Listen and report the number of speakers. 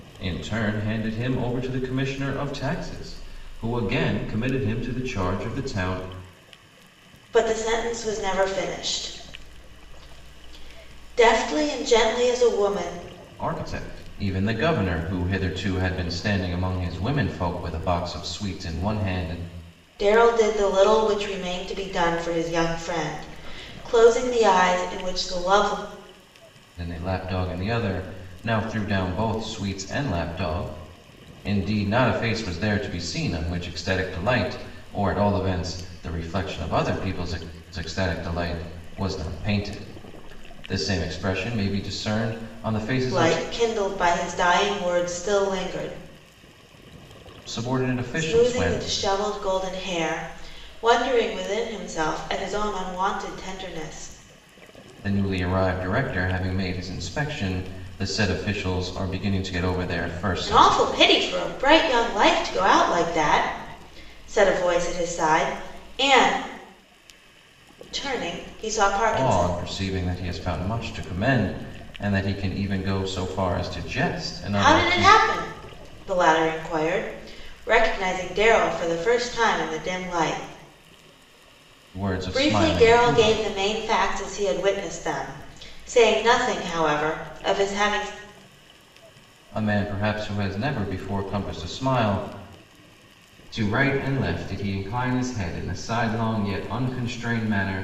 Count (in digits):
2